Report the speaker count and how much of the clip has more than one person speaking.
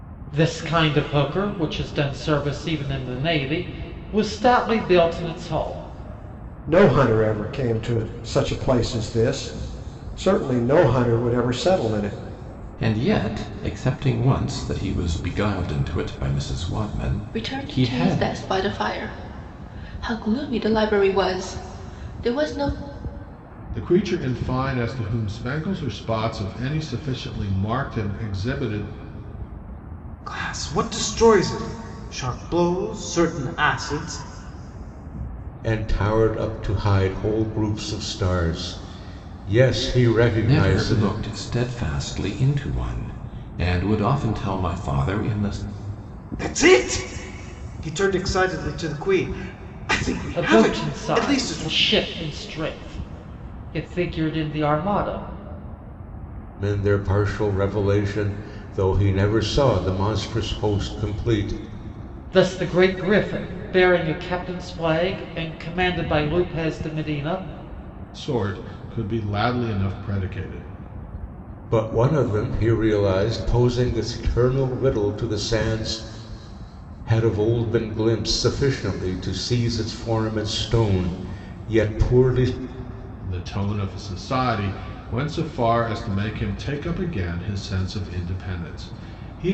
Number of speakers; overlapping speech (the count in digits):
7, about 4%